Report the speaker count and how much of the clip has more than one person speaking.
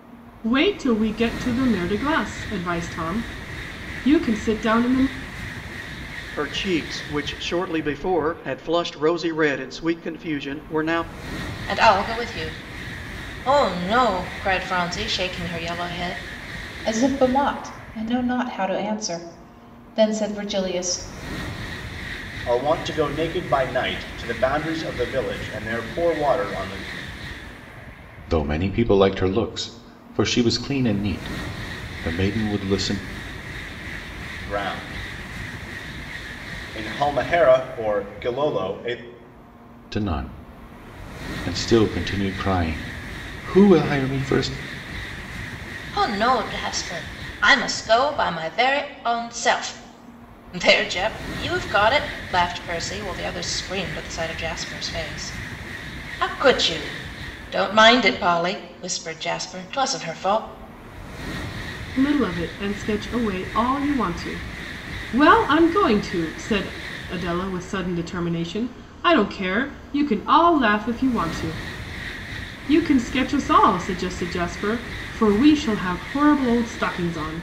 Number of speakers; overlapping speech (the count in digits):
6, no overlap